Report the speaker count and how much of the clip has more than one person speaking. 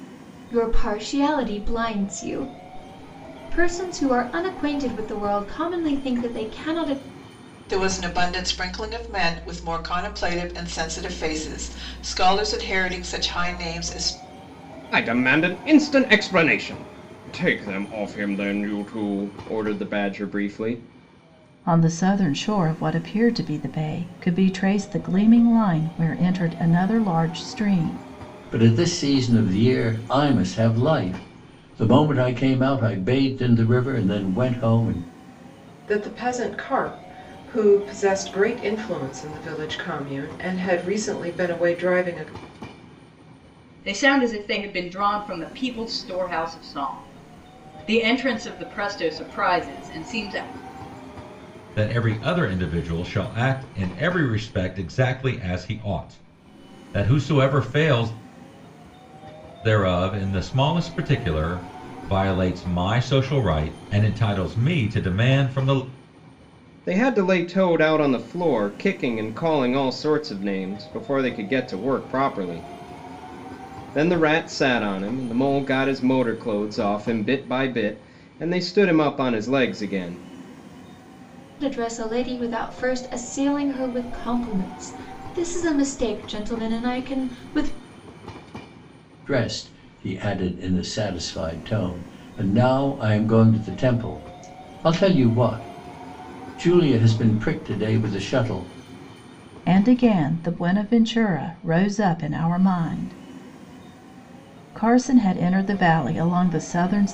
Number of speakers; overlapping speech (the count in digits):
8, no overlap